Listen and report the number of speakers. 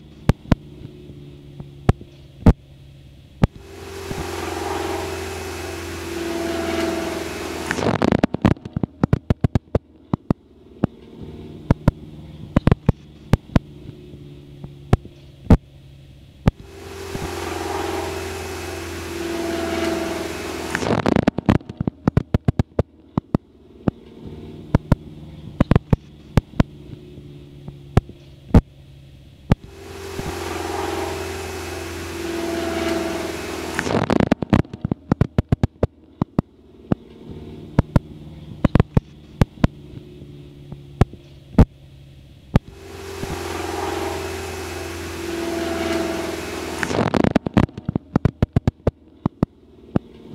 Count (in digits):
0